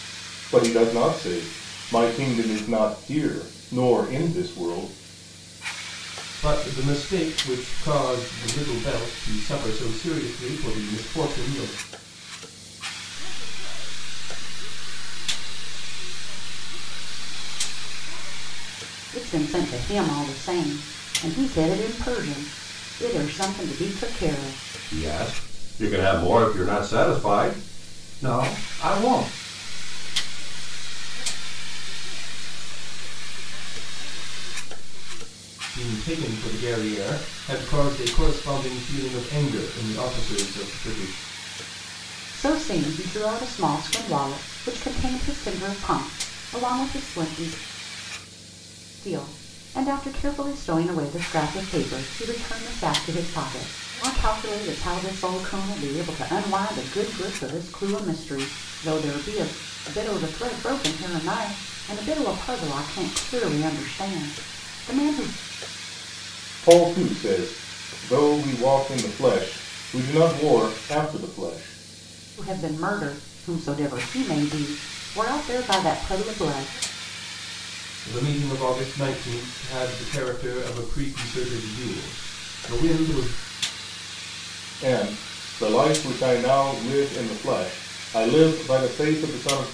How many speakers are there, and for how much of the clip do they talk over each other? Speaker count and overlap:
five, no overlap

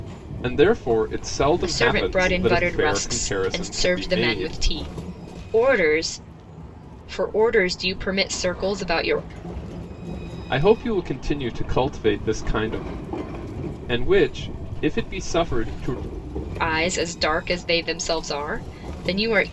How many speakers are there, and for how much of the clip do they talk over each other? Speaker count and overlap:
two, about 16%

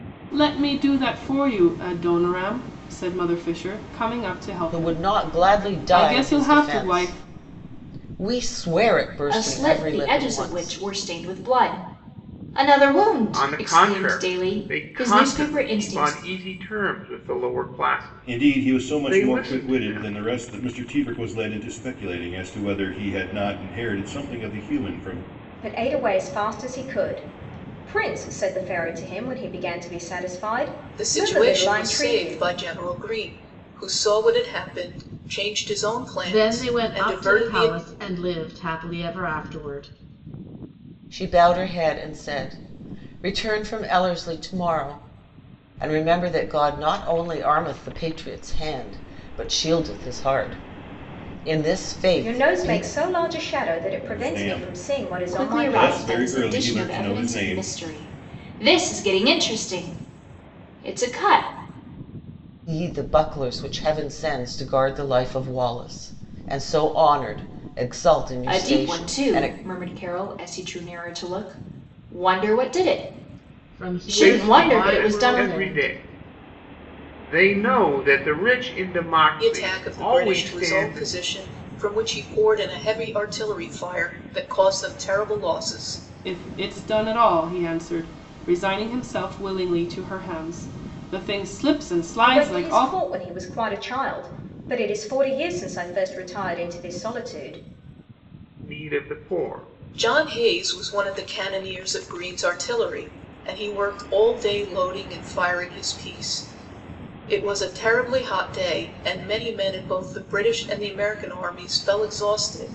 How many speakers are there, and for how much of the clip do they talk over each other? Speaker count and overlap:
eight, about 20%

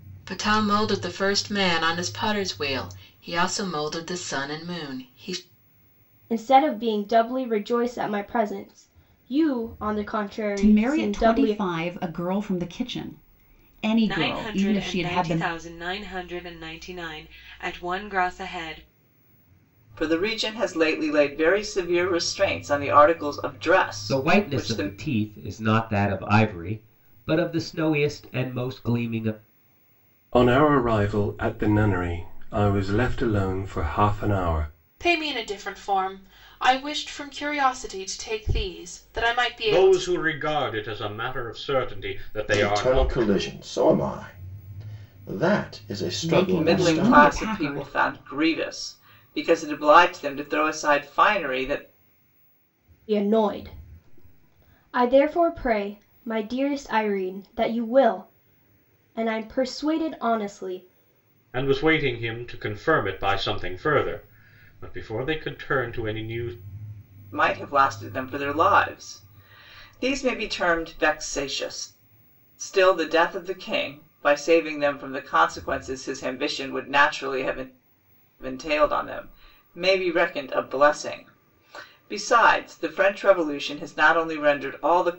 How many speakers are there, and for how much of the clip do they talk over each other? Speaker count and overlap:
ten, about 8%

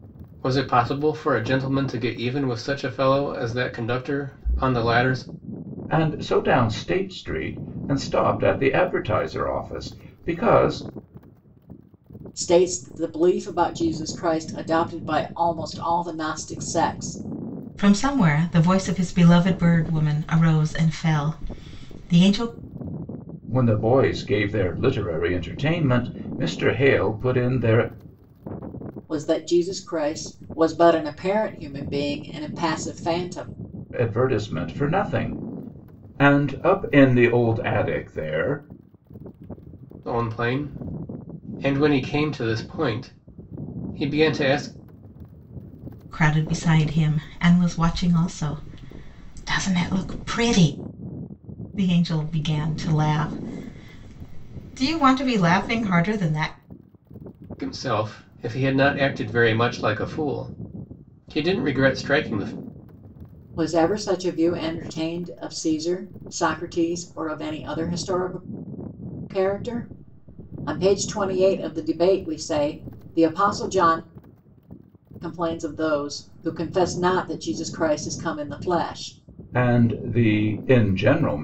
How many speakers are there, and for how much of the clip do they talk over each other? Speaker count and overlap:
four, no overlap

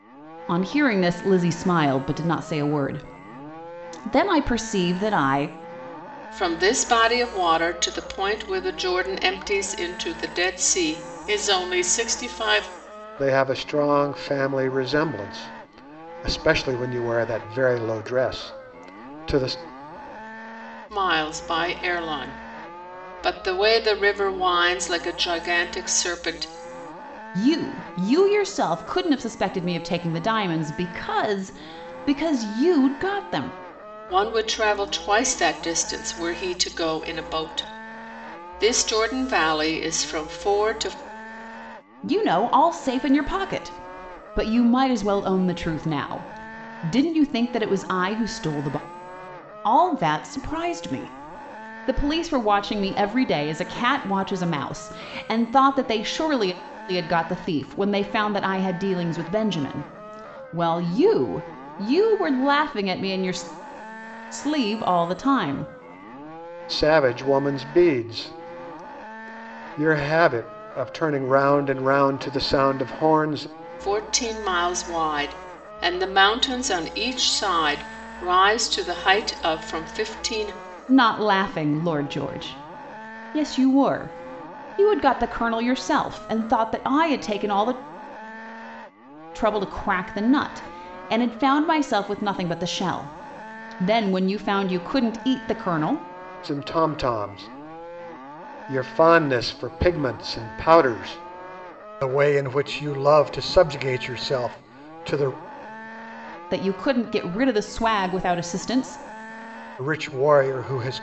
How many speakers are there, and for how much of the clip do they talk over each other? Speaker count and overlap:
three, no overlap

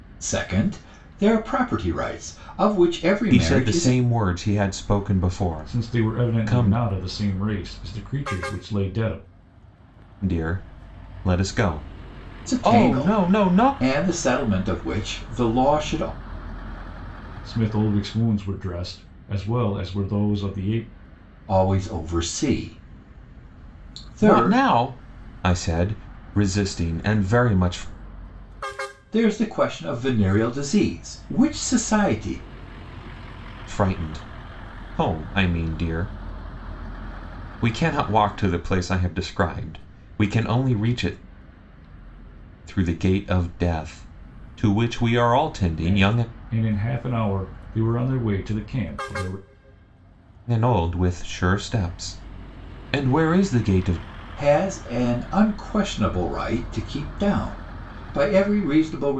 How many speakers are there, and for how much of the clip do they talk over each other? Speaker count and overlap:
three, about 7%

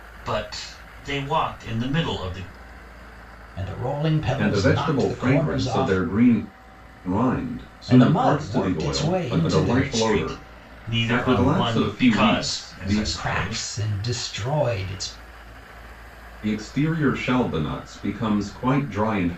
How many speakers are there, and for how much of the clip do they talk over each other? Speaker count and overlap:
three, about 35%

